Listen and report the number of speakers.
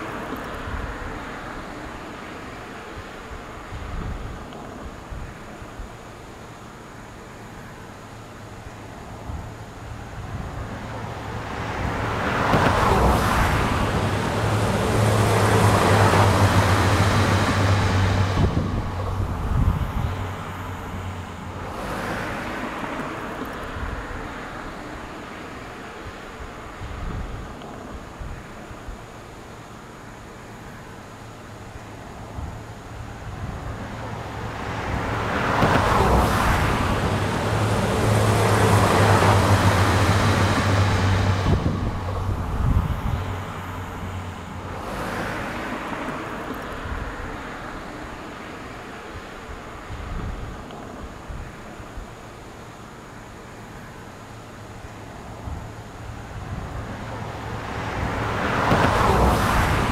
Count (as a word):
zero